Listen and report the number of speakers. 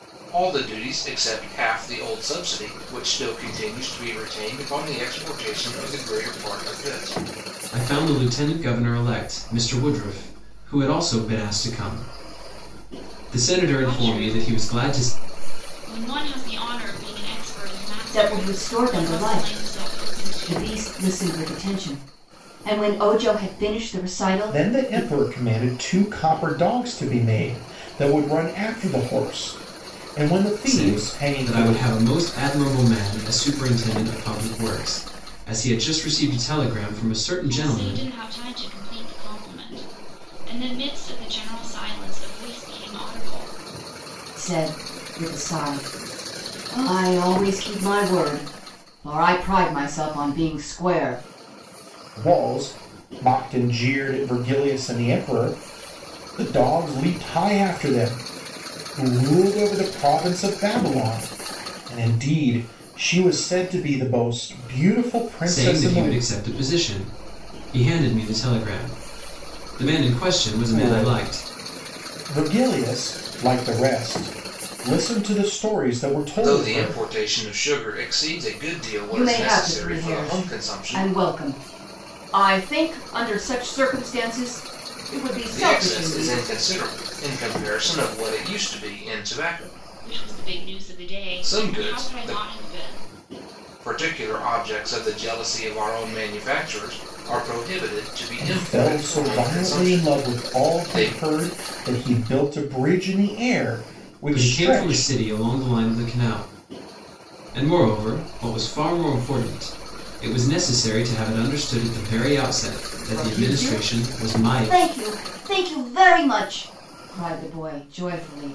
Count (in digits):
5